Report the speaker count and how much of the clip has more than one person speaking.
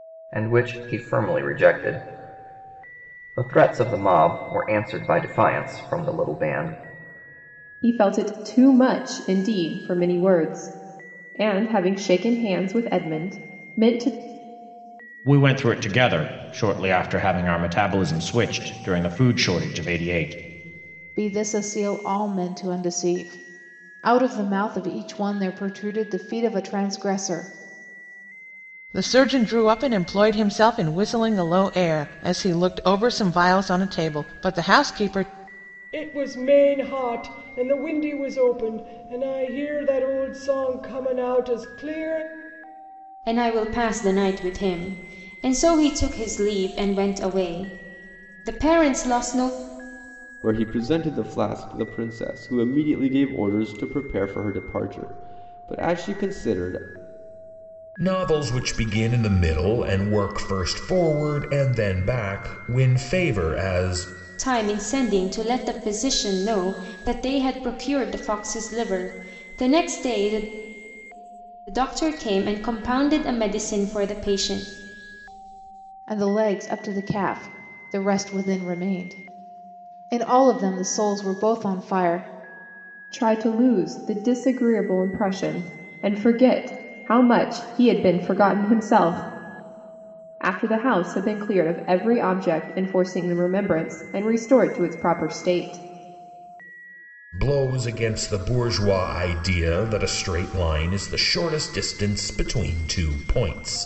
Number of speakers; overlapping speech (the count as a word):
nine, no overlap